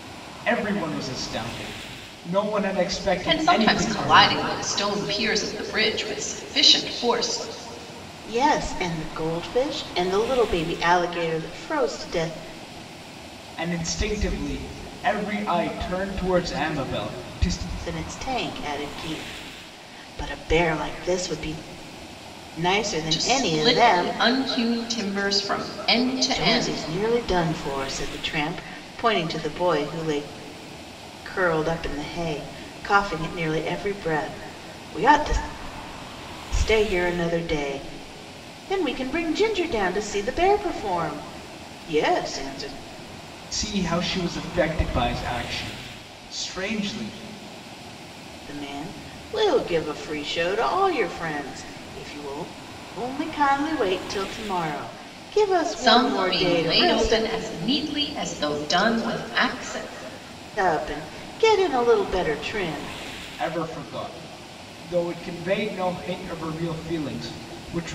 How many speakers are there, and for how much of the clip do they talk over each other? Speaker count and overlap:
three, about 6%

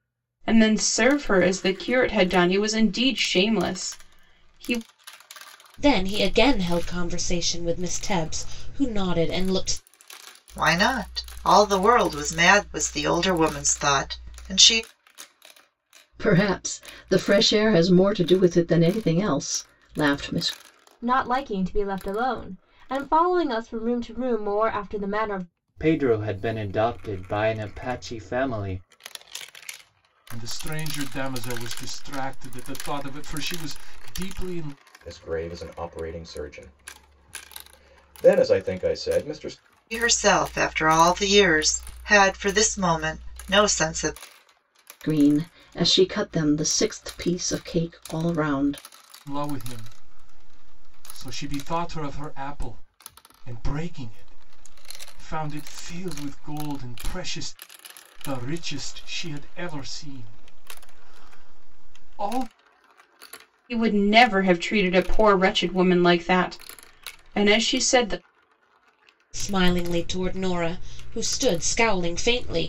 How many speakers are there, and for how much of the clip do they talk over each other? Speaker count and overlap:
eight, no overlap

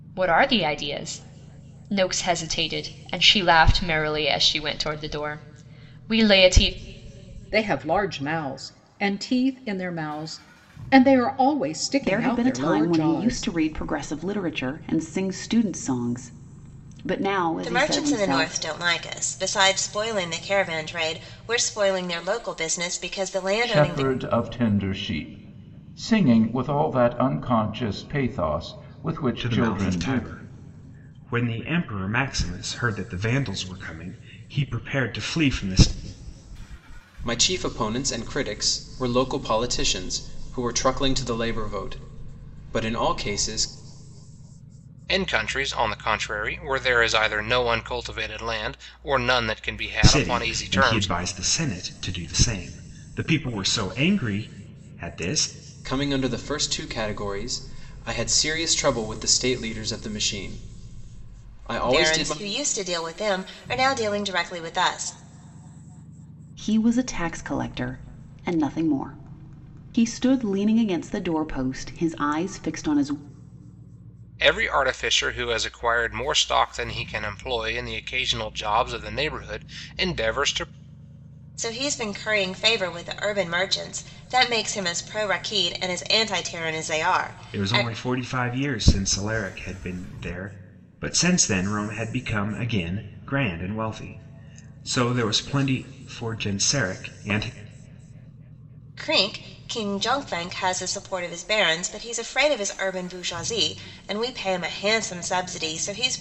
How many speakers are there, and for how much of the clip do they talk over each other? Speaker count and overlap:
eight, about 6%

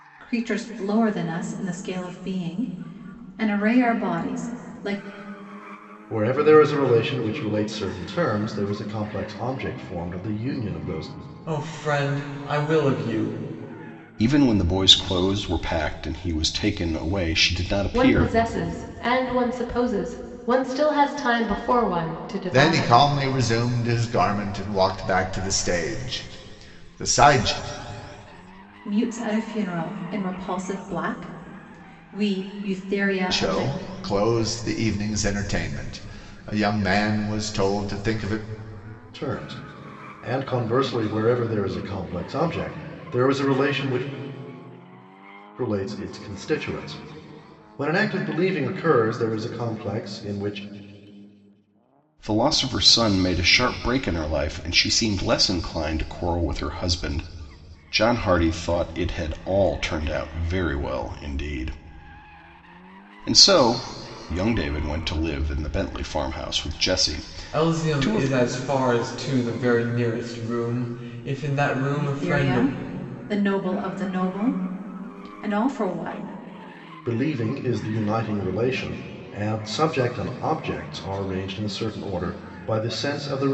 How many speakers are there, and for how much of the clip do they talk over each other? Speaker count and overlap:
six, about 4%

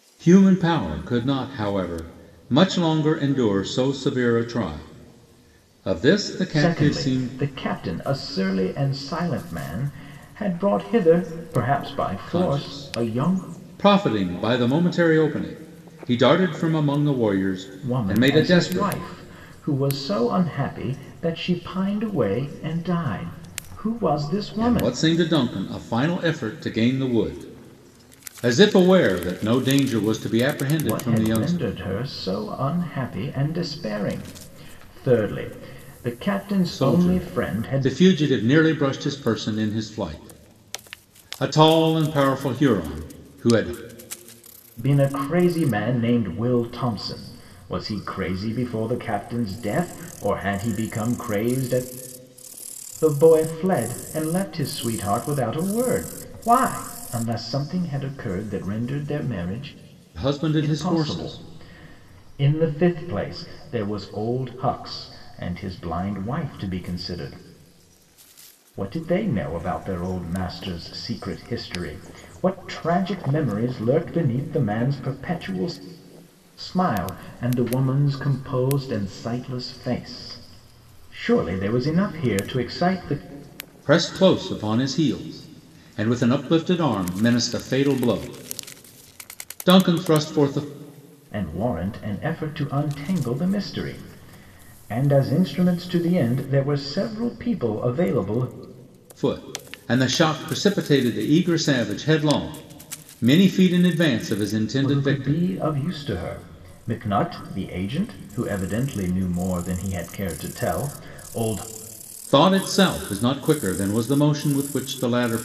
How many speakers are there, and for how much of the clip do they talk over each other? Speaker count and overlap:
two, about 6%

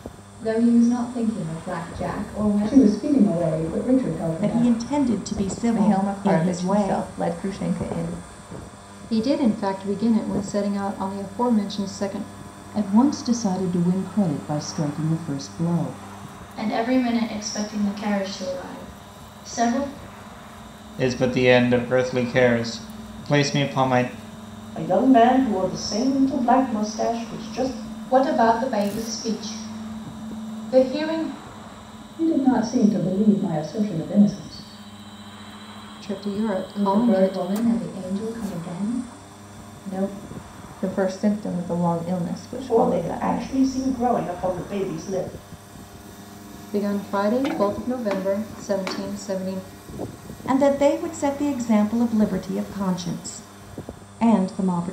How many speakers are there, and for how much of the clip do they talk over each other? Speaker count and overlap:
ten, about 8%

